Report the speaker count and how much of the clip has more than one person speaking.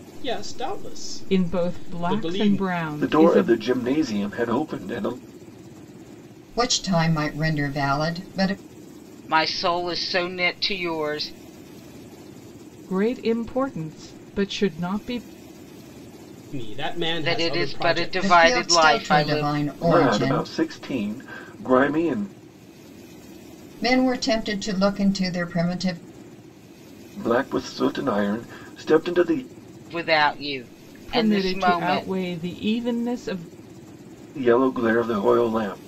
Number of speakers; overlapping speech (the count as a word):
five, about 17%